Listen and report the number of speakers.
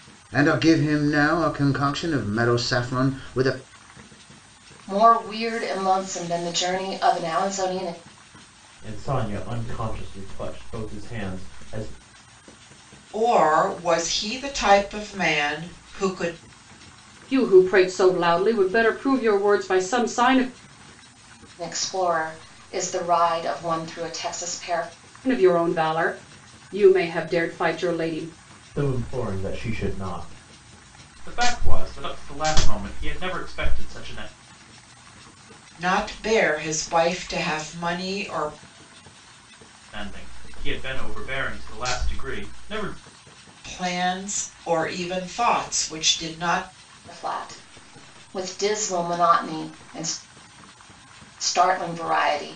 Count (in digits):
5